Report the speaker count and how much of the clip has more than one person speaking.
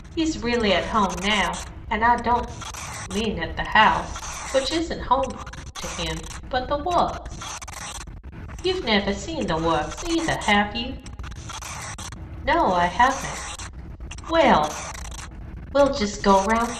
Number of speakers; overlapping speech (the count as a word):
one, no overlap